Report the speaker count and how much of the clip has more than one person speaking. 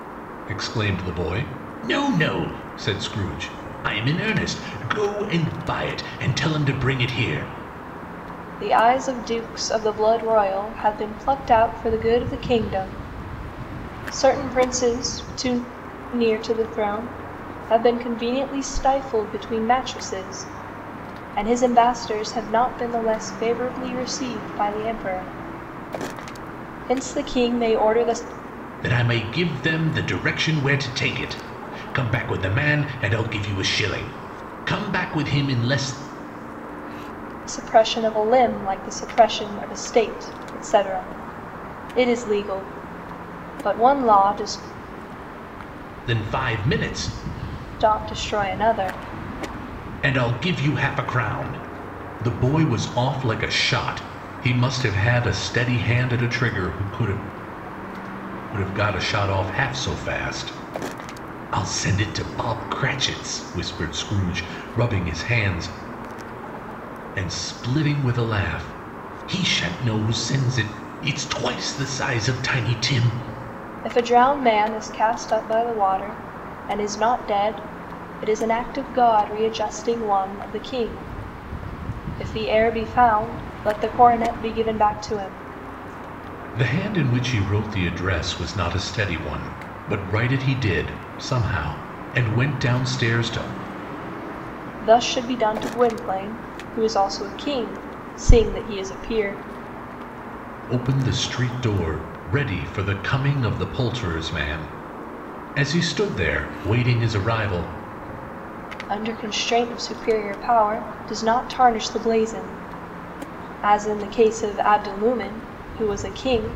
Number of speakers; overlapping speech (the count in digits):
2, no overlap